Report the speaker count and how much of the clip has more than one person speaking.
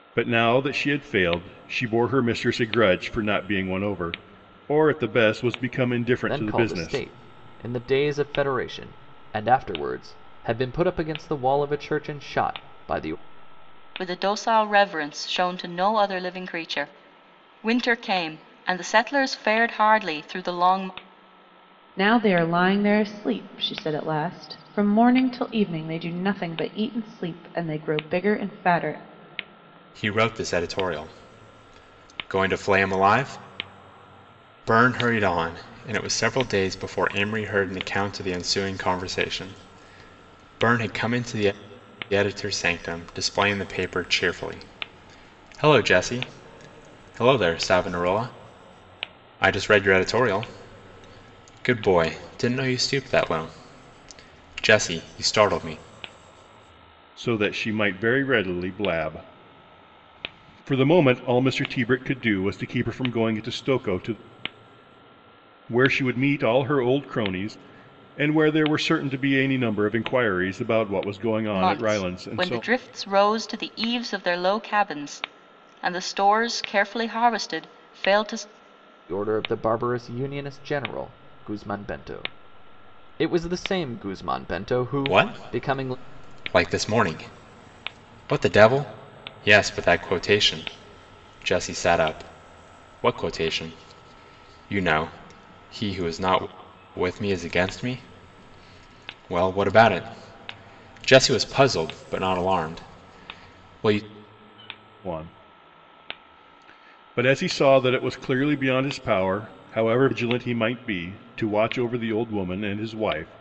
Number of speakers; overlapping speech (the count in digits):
5, about 3%